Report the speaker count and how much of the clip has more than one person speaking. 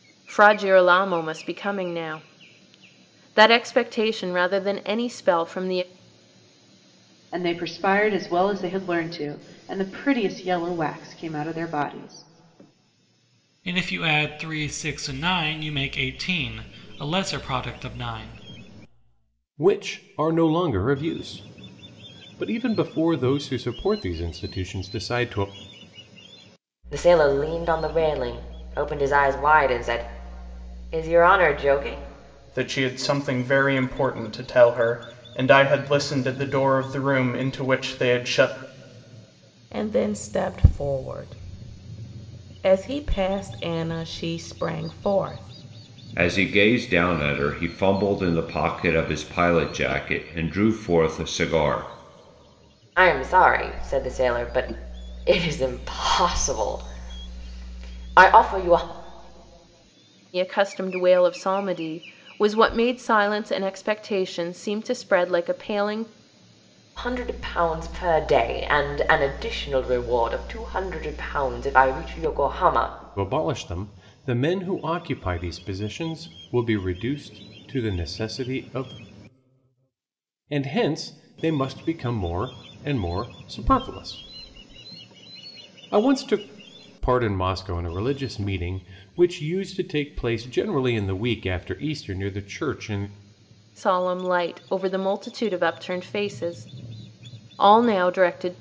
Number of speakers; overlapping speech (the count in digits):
8, no overlap